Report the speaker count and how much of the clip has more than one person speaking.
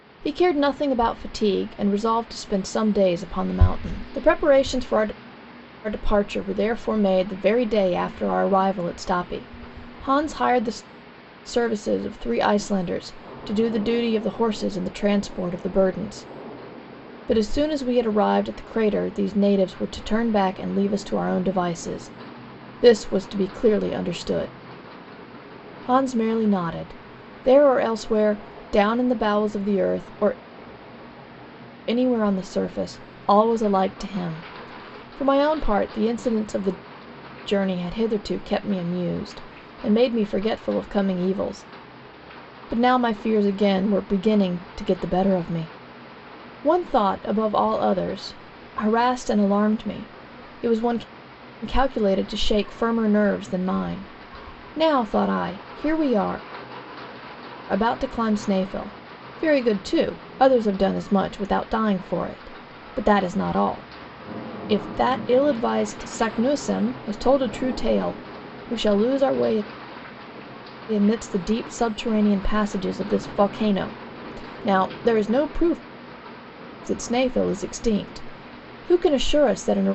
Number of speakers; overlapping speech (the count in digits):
1, no overlap